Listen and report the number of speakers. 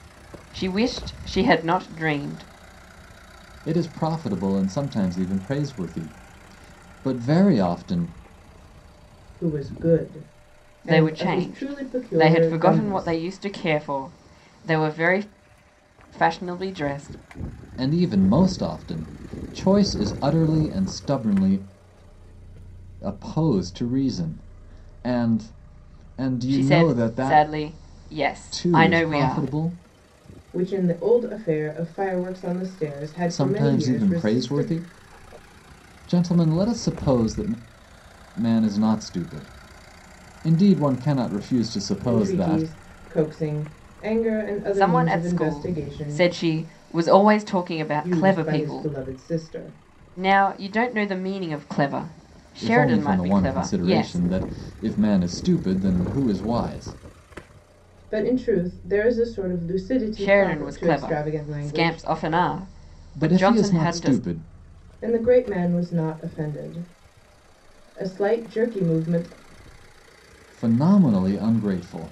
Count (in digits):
3